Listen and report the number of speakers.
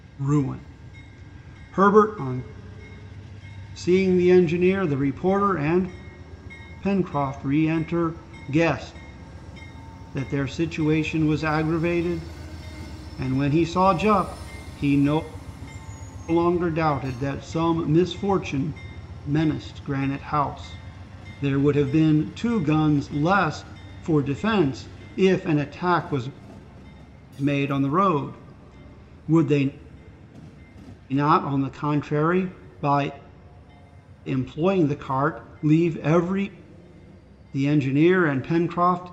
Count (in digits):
1